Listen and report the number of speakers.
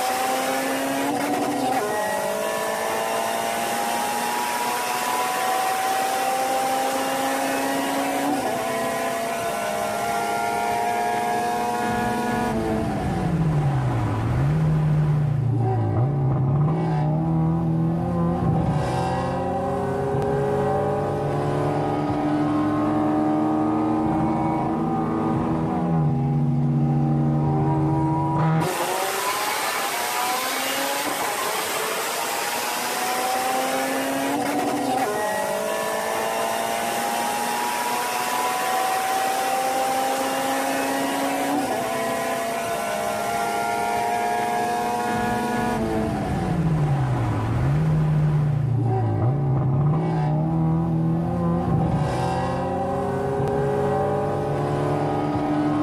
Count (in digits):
0